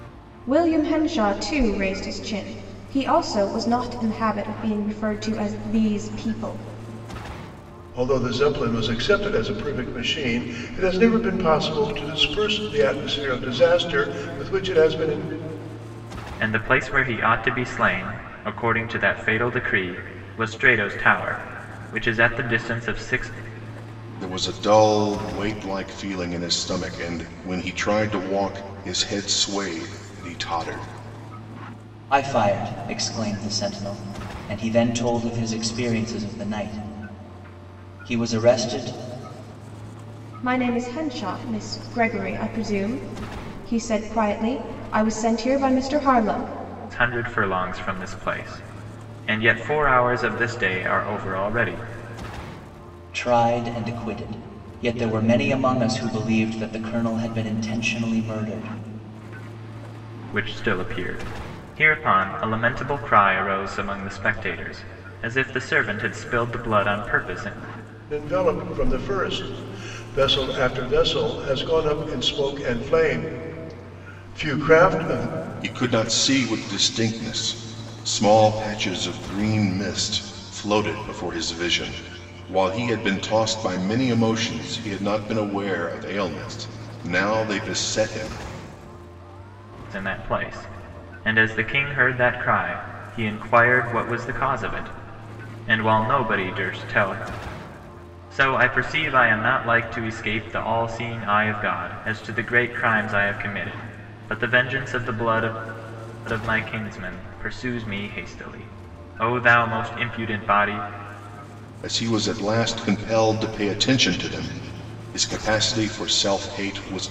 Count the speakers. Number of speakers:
5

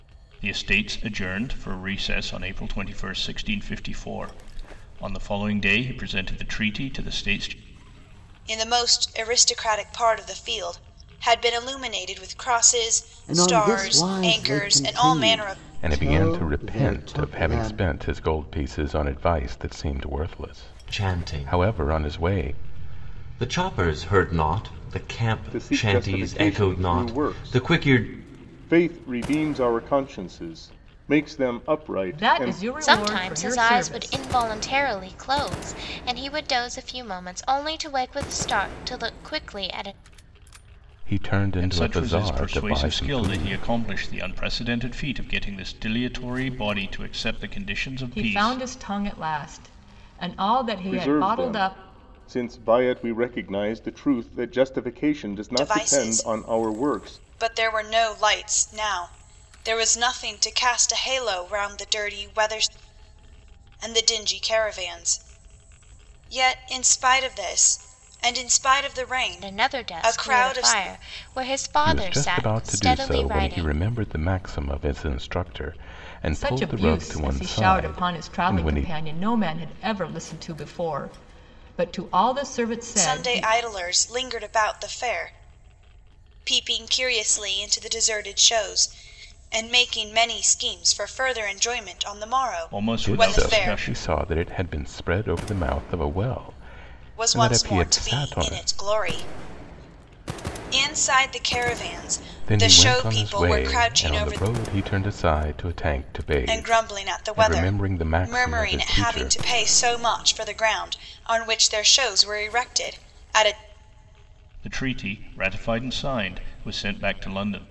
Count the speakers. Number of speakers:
8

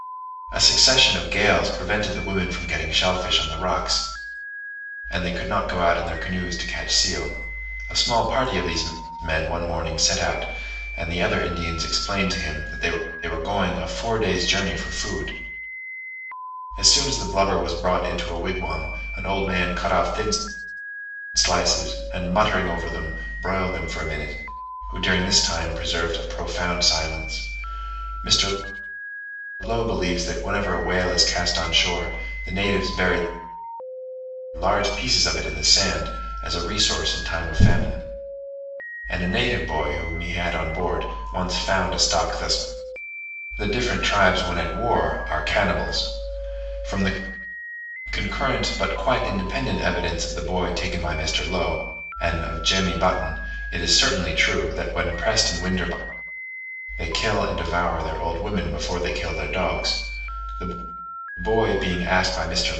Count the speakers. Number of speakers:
1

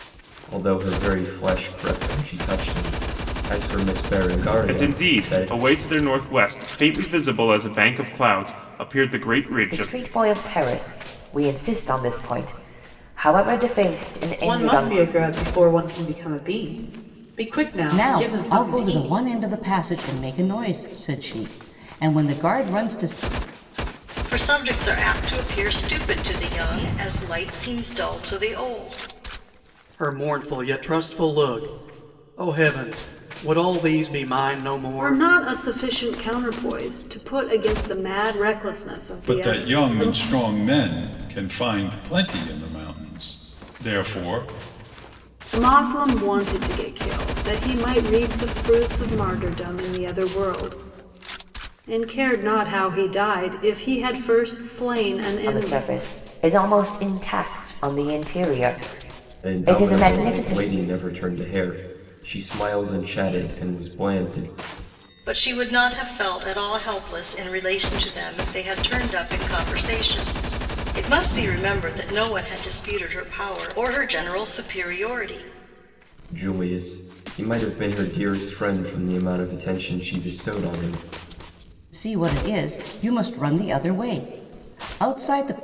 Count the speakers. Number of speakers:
9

